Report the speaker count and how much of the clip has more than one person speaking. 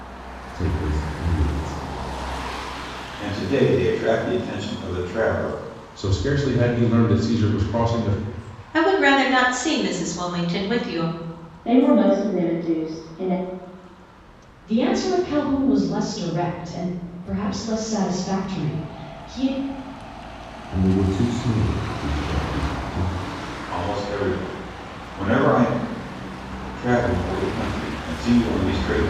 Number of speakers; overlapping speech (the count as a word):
six, no overlap